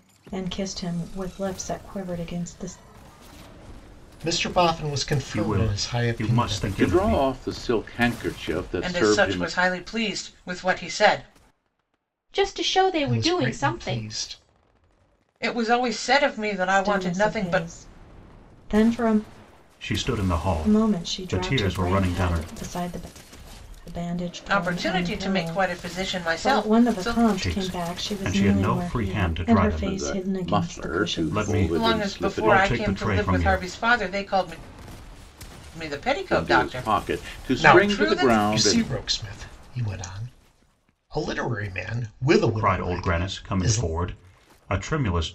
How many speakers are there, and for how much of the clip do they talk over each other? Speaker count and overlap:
6, about 43%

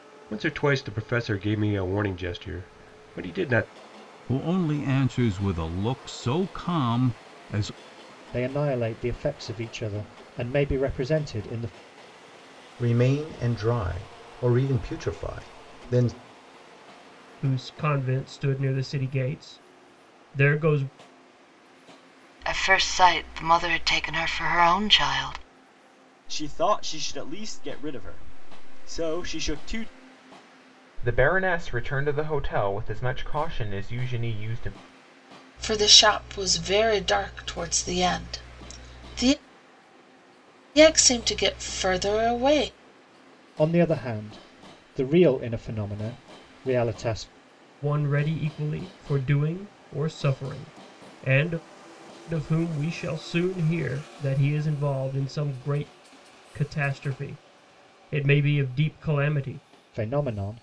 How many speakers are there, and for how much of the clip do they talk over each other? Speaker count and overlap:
9, no overlap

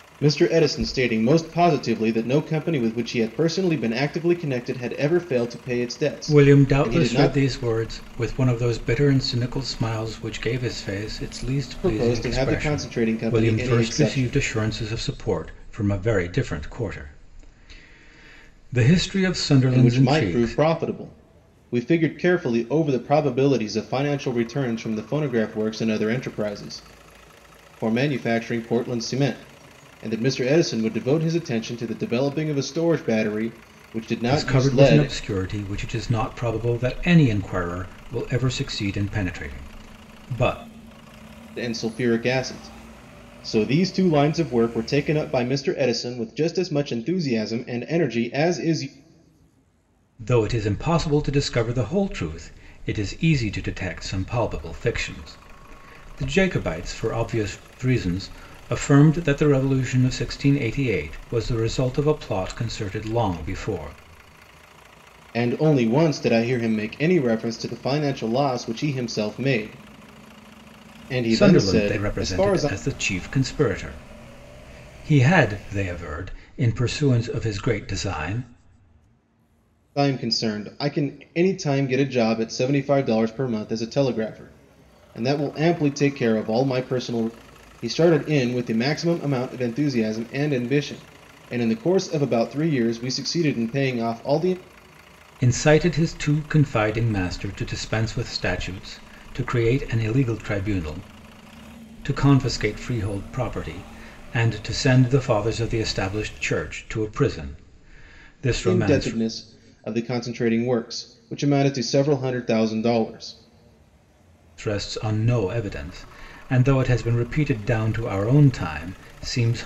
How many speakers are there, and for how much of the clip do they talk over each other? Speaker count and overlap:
2, about 6%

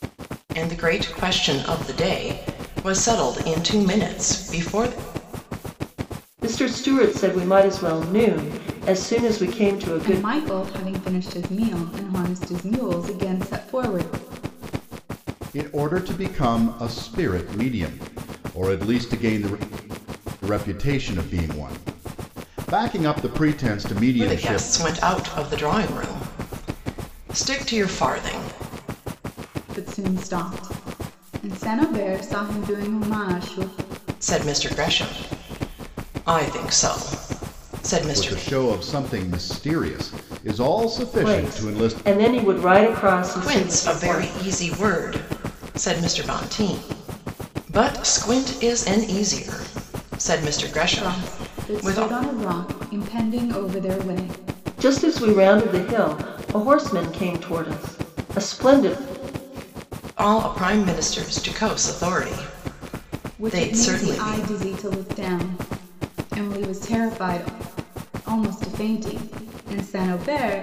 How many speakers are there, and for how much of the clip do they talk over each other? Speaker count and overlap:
4, about 8%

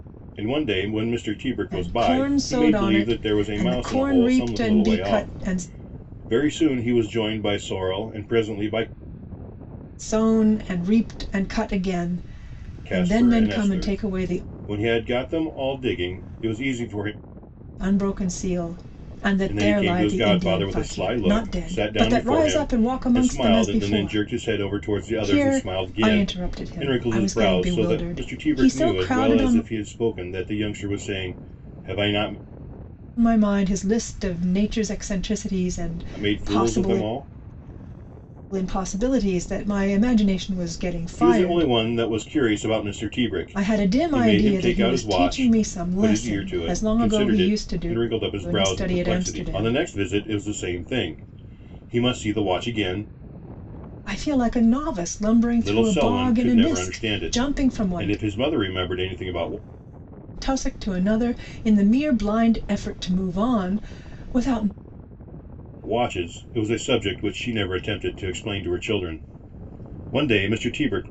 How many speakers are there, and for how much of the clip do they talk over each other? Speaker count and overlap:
2, about 34%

